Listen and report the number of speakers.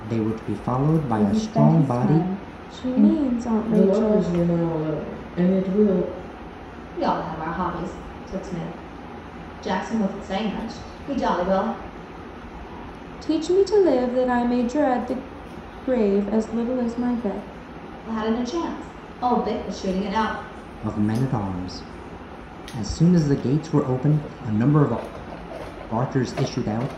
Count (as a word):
five